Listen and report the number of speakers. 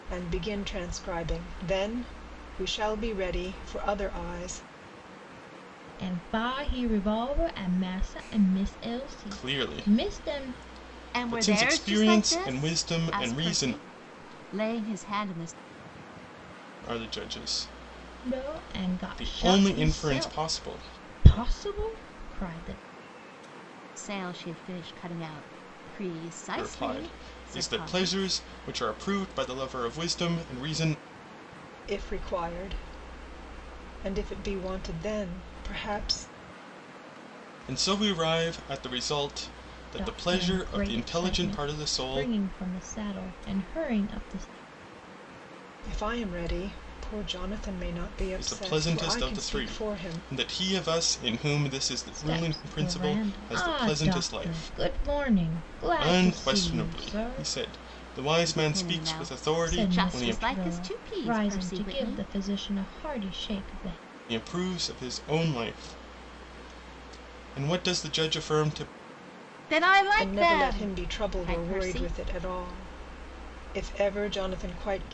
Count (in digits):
4